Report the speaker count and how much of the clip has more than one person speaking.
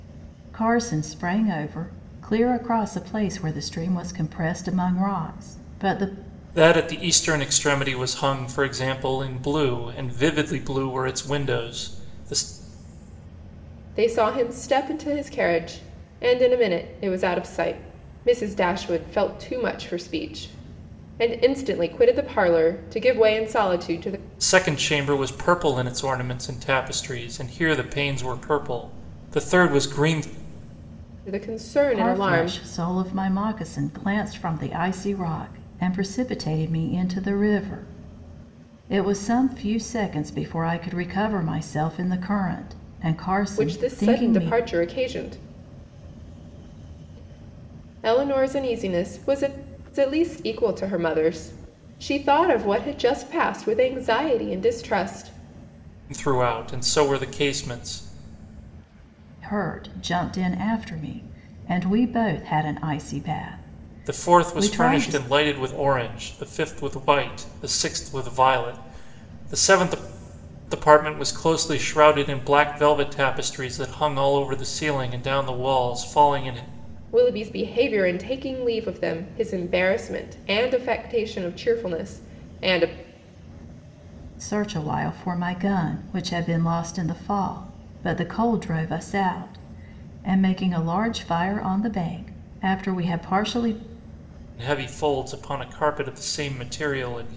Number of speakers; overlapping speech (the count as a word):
three, about 3%